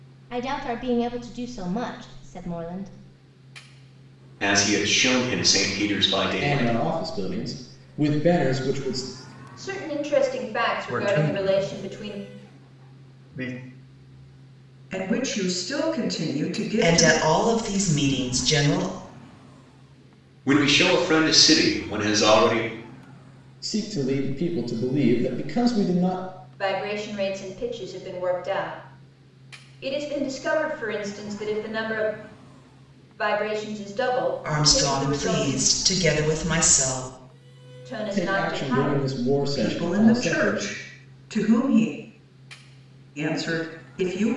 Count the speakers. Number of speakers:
seven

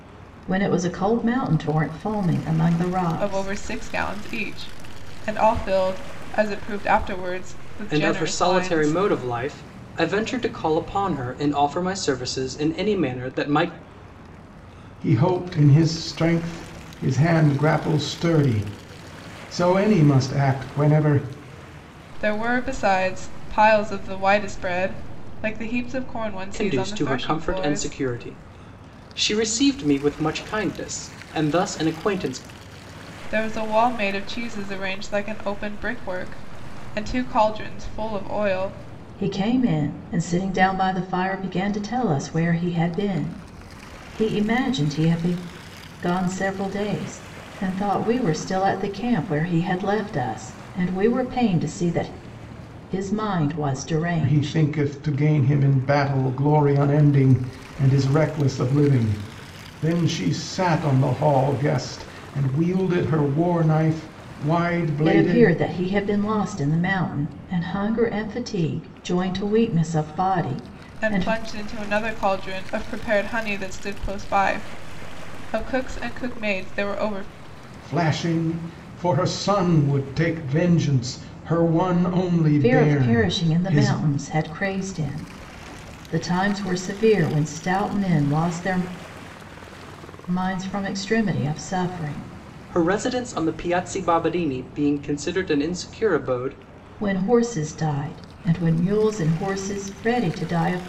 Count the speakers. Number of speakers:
four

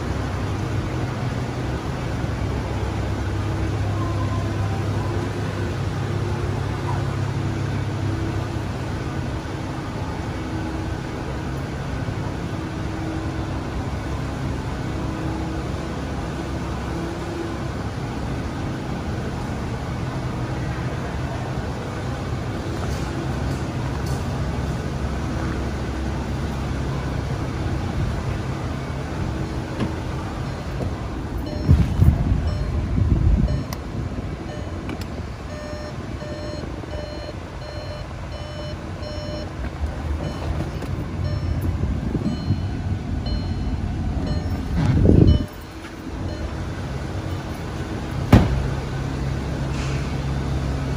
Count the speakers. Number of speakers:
zero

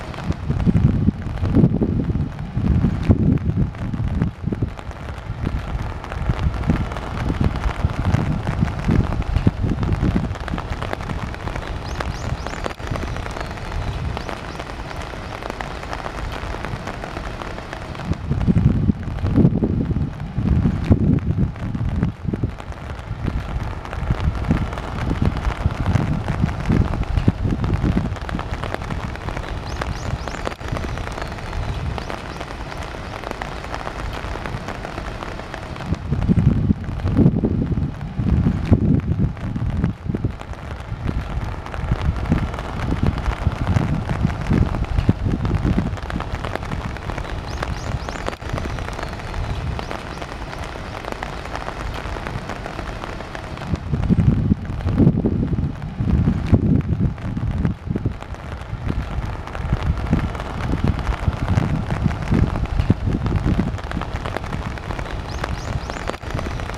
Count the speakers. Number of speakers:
zero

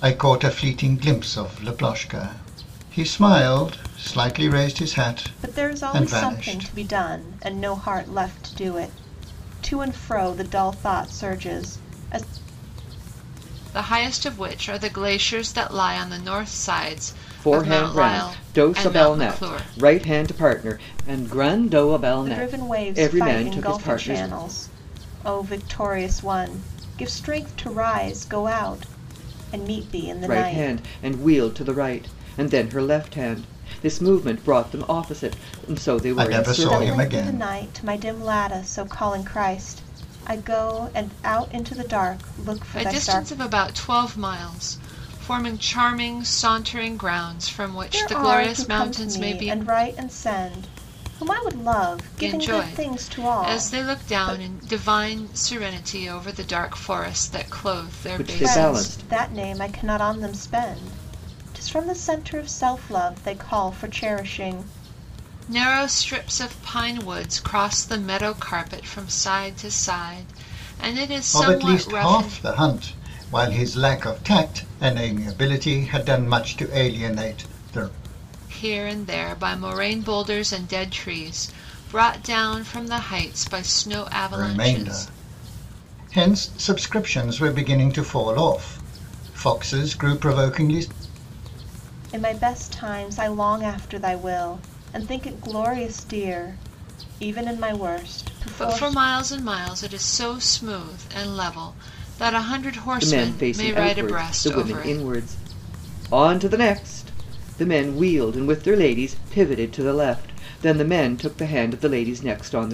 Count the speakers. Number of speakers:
four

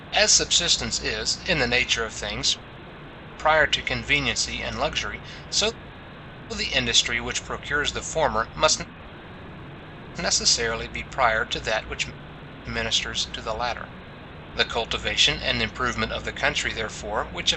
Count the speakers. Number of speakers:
one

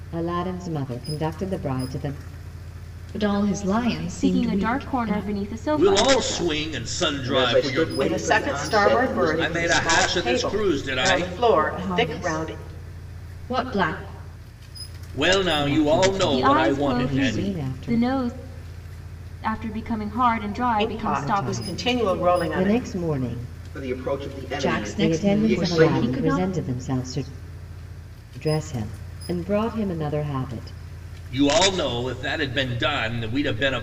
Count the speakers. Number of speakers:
six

